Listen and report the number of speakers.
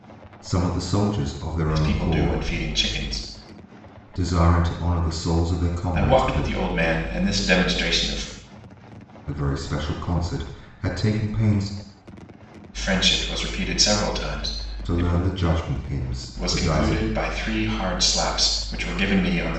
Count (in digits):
2